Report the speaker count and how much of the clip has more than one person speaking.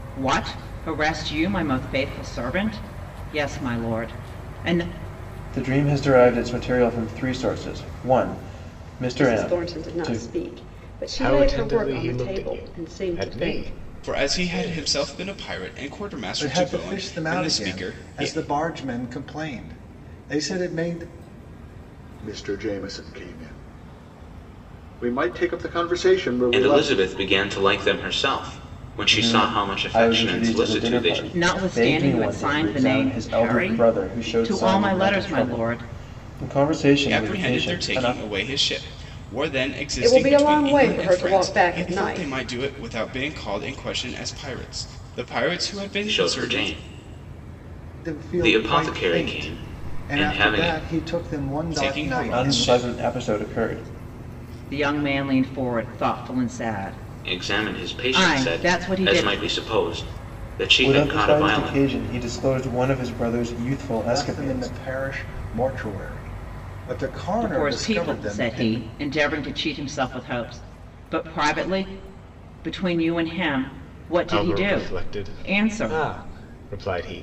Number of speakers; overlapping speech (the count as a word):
eight, about 38%